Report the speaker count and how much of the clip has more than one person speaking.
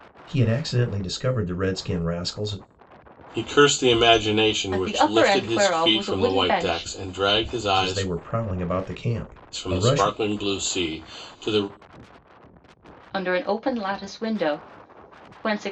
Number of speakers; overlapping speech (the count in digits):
3, about 20%